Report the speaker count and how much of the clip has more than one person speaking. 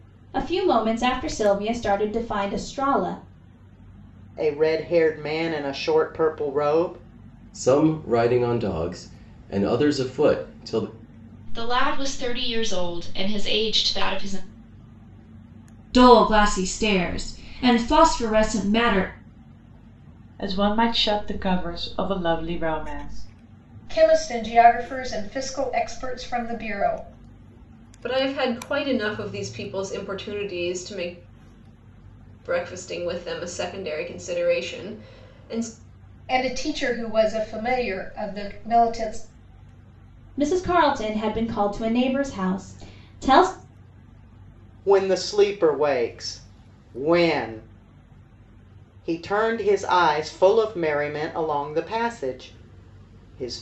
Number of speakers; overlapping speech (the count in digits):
8, no overlap